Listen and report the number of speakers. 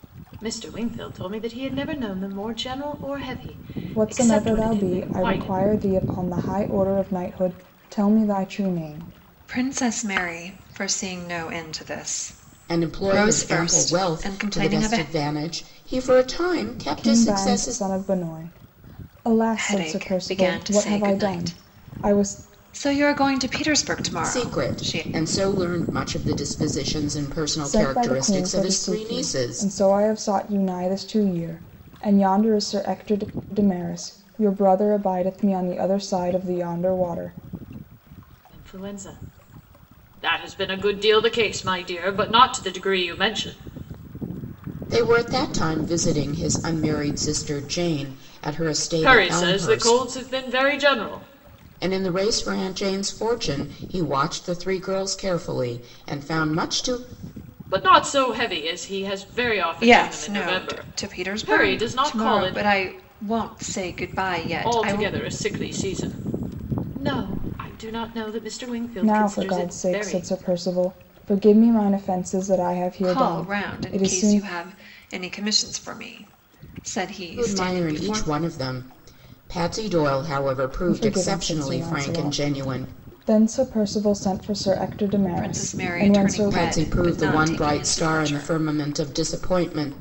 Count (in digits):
4